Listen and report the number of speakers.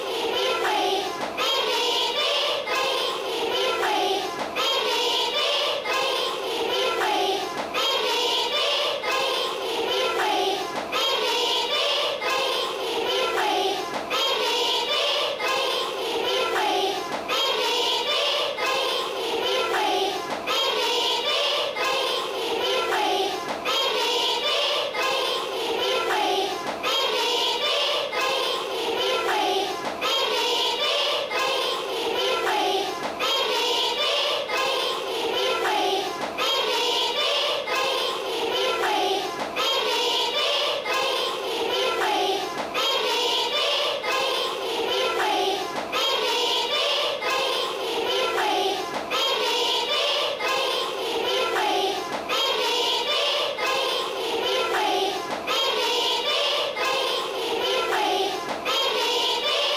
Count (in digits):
0